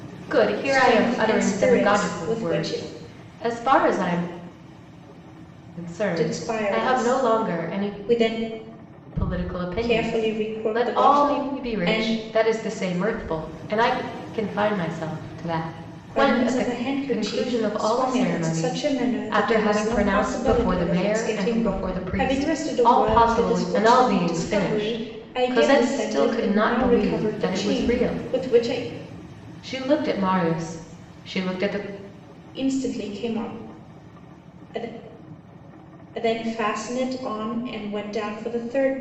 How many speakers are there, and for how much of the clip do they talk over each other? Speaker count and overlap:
2, about 46%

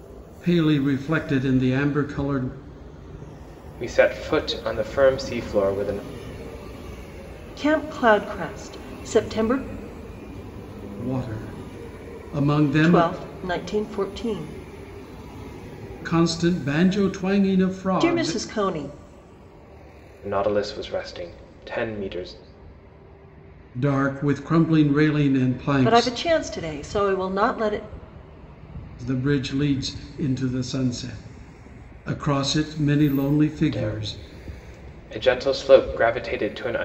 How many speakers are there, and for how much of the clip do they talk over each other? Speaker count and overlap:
3, about 4%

